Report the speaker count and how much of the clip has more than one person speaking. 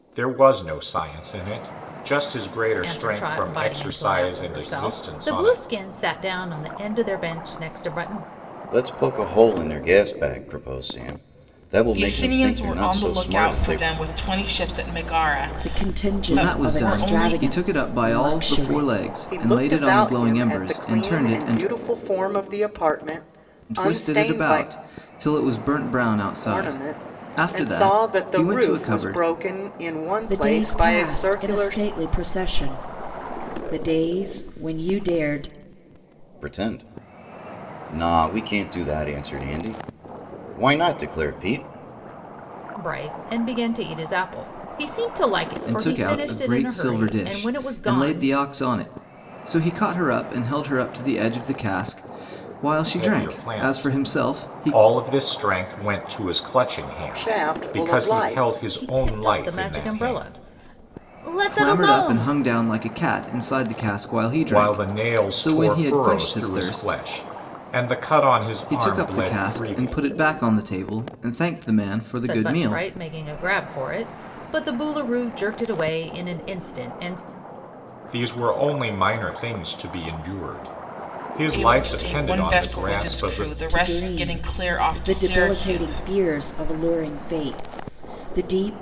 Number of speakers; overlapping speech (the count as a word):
seven, about 38%